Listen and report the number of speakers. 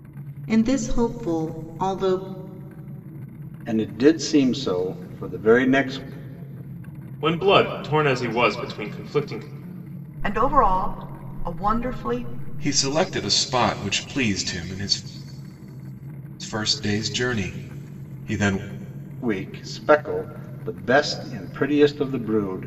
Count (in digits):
5